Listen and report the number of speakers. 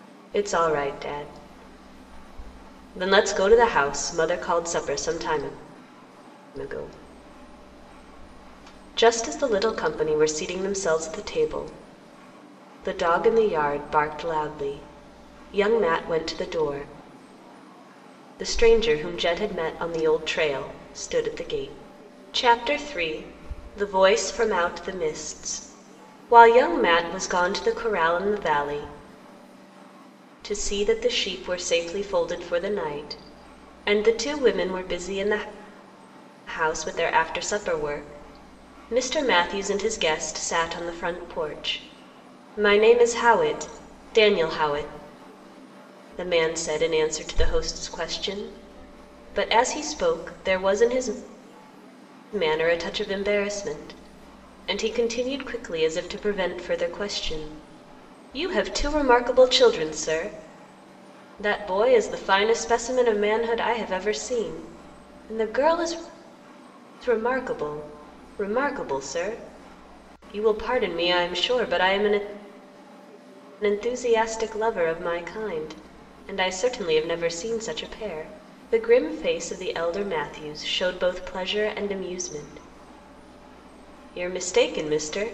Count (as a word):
one